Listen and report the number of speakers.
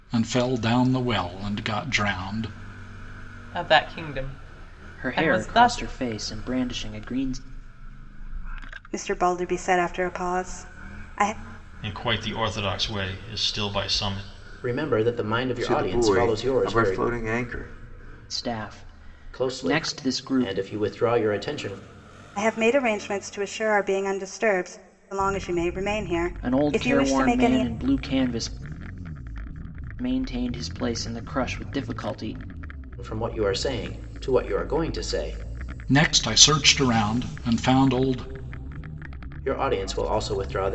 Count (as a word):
seven